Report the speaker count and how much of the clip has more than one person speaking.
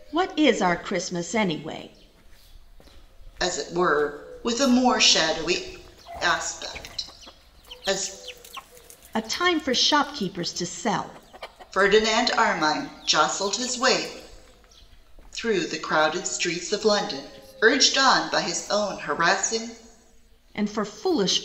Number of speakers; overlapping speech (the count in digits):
2, no overlap